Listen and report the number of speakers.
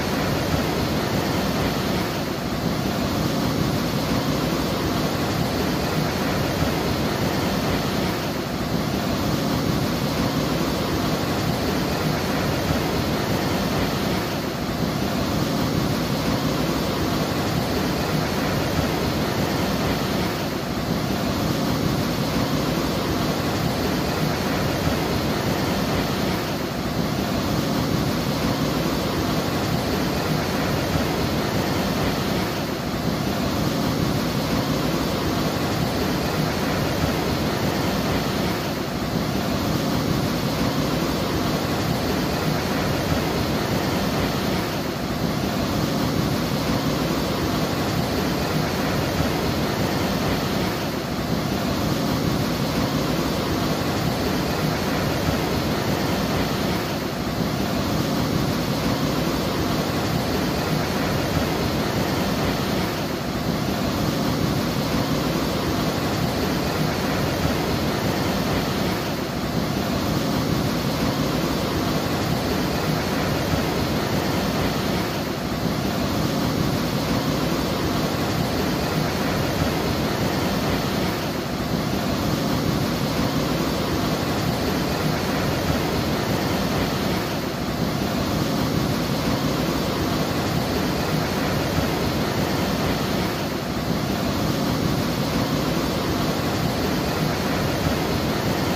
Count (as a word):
zero